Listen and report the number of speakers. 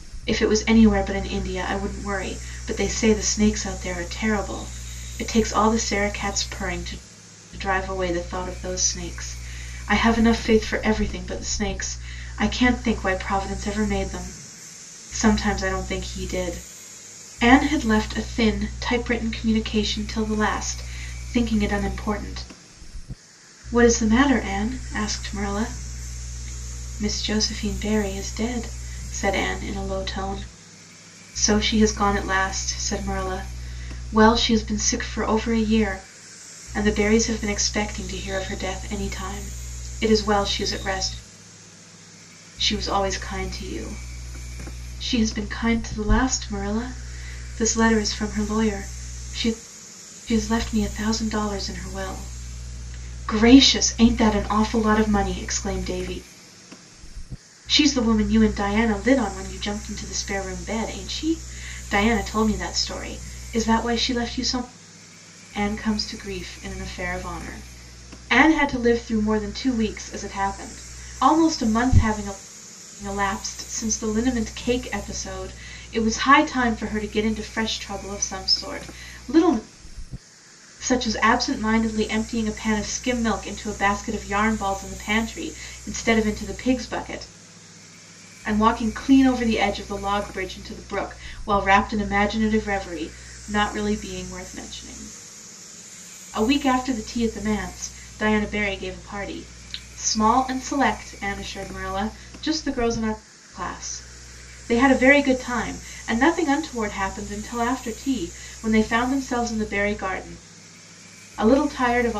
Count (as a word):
one